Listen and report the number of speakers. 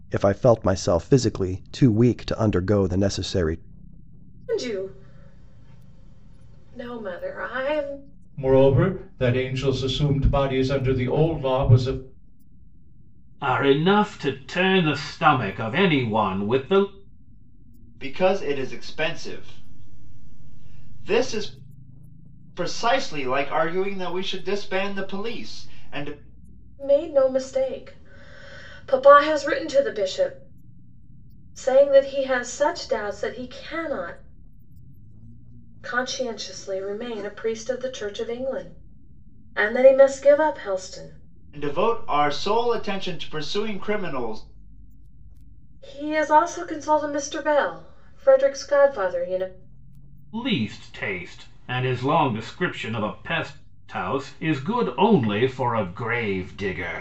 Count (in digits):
5